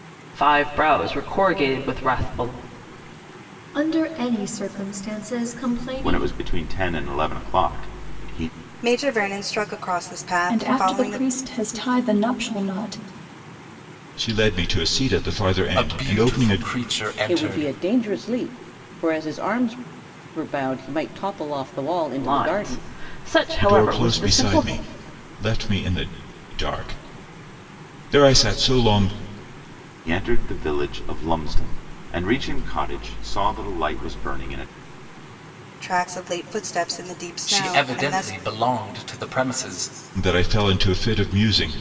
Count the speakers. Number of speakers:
8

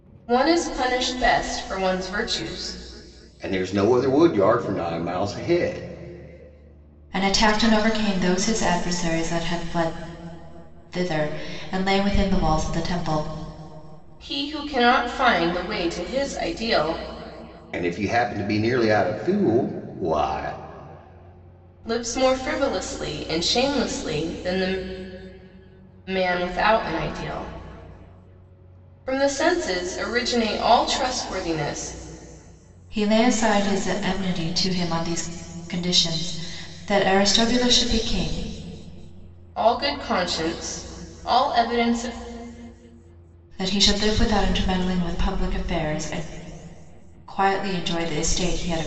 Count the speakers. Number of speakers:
3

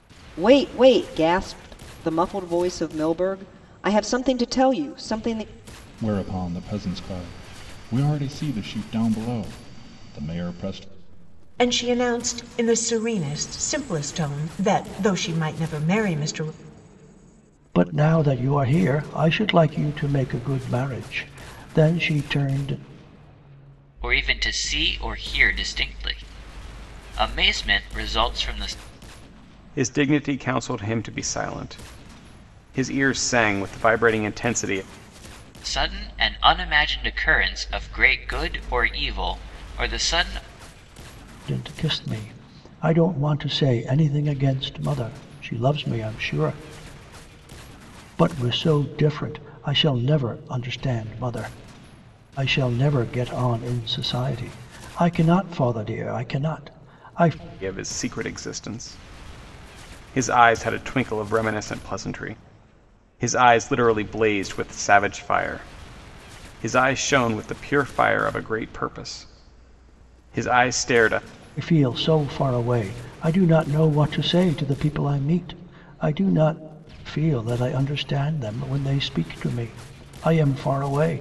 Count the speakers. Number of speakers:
6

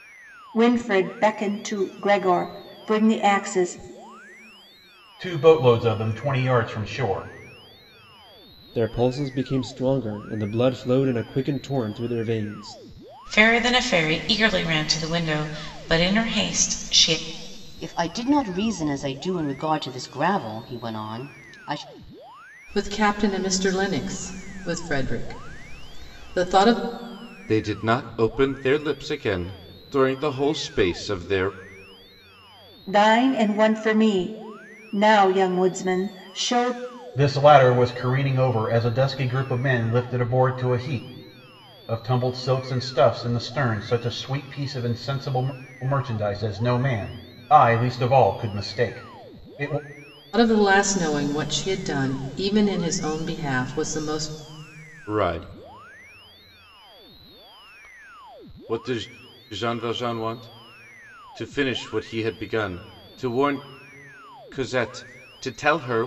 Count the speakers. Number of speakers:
7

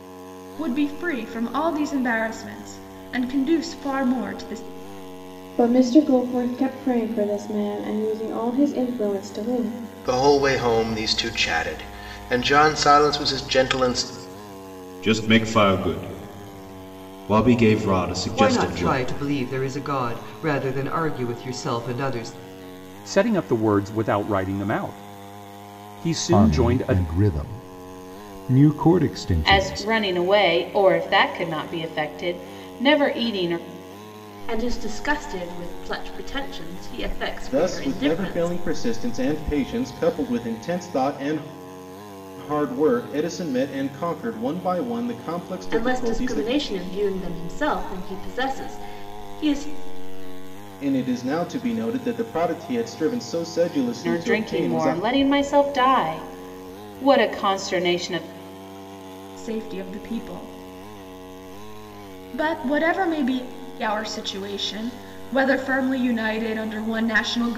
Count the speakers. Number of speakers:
10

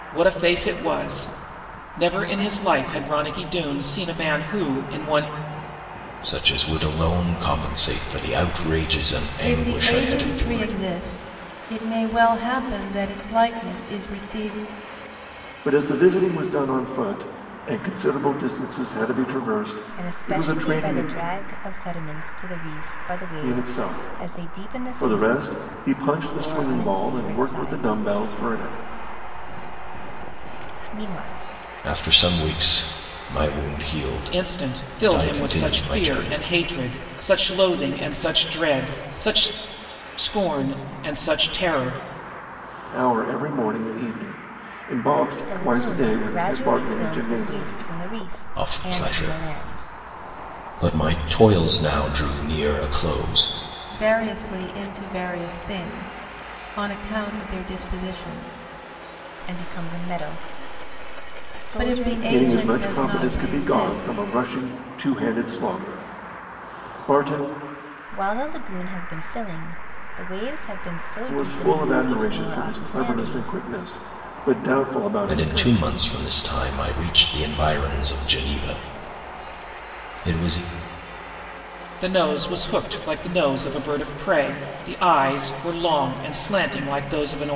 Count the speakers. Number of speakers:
5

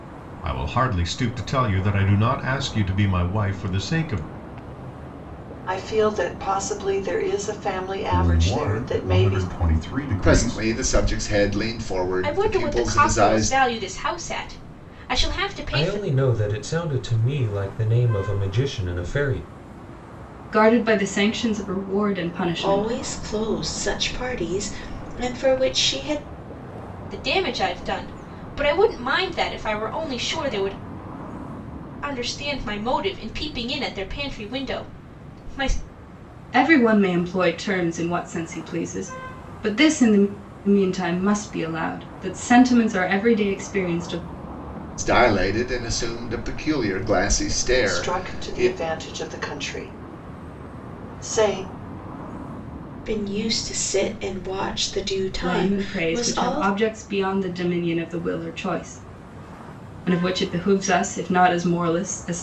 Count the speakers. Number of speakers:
8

